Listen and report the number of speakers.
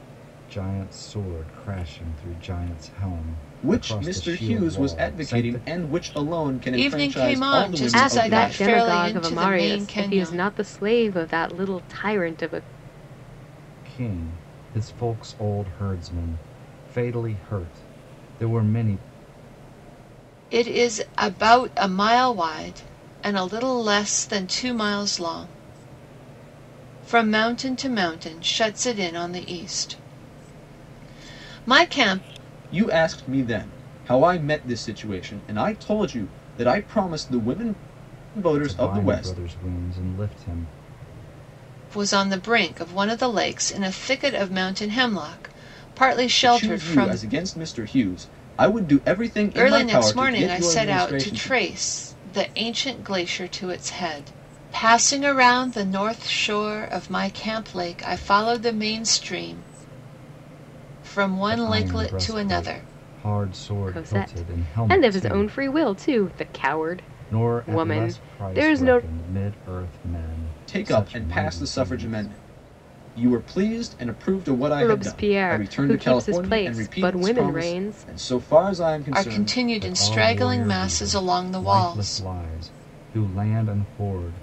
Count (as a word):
four